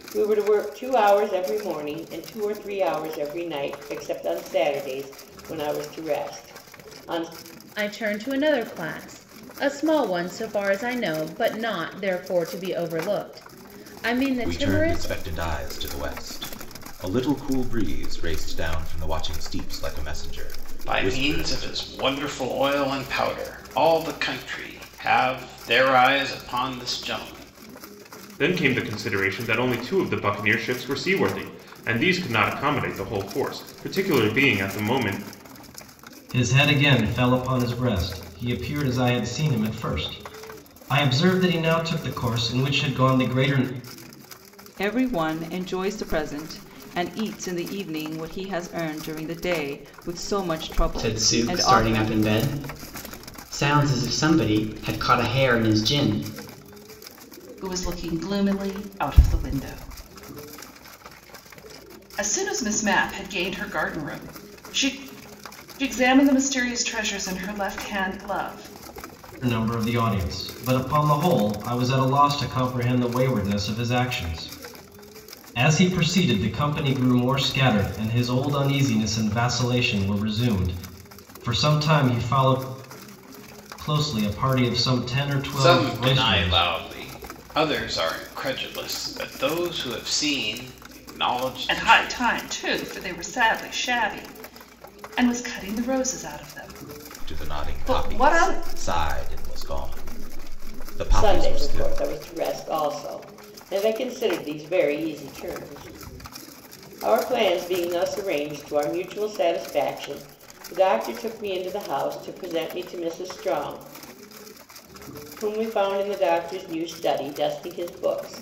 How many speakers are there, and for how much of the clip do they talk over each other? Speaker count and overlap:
nine, about 6%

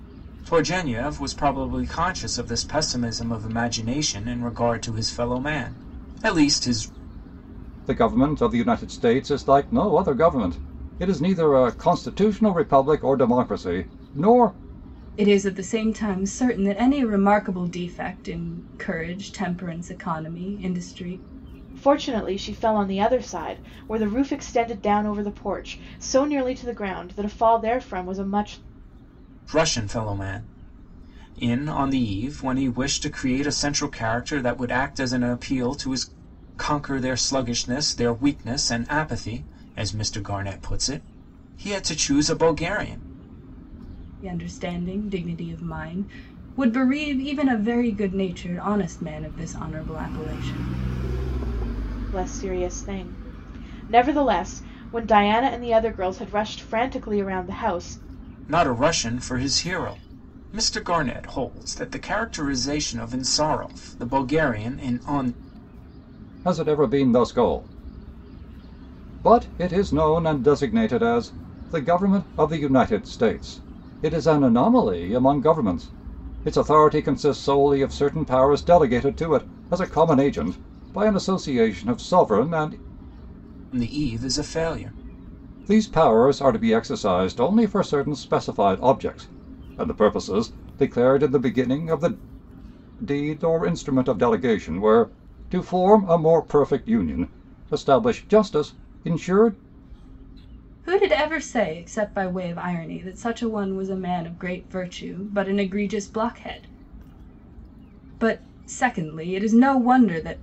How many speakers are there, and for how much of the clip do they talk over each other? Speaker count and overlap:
four, no overlap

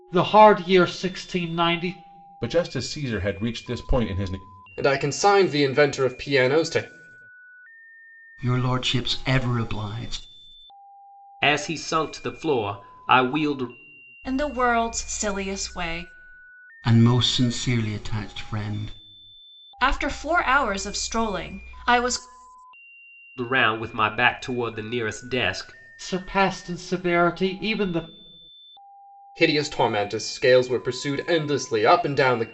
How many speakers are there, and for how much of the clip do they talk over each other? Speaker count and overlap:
six, no overlap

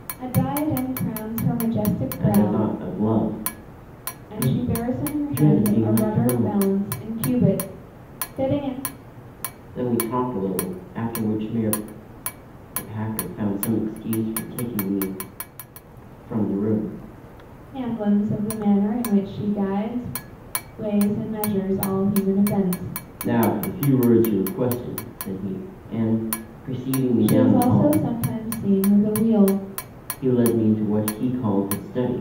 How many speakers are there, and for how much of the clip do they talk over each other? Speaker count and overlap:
two, about 9%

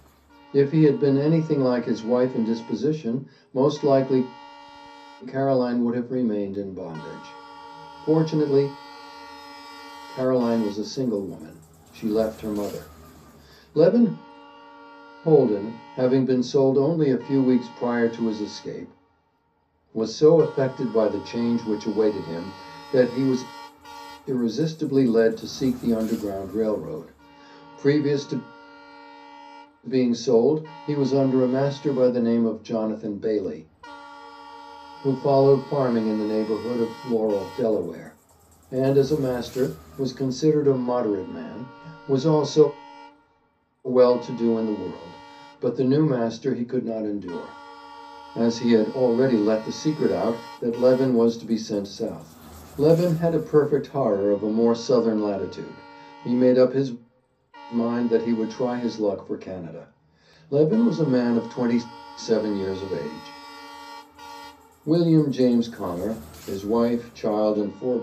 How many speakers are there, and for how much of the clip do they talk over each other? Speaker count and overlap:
one, no overlap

